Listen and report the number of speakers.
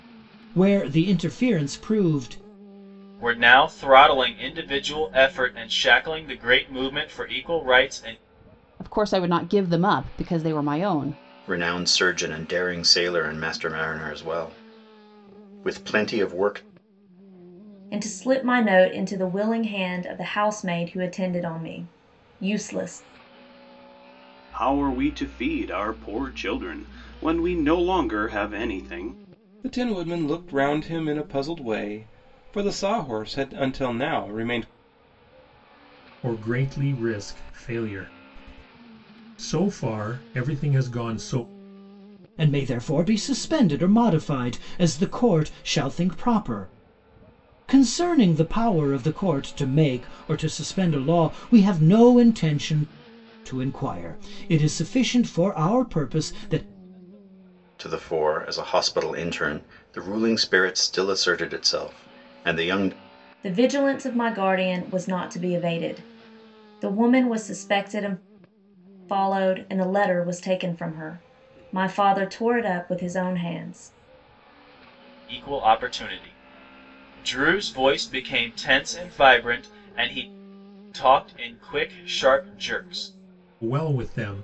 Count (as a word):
eight